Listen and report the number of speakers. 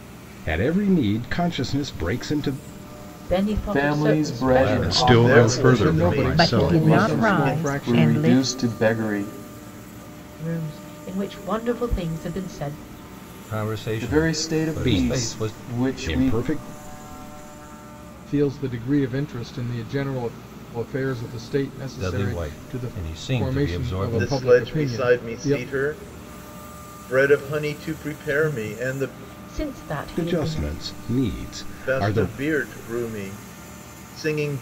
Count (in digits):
8